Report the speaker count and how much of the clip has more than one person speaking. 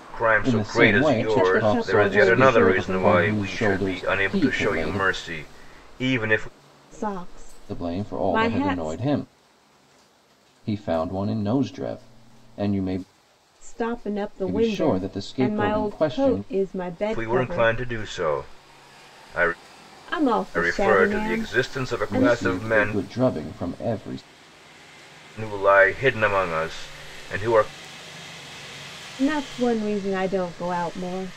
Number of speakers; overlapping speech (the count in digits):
3, about 35%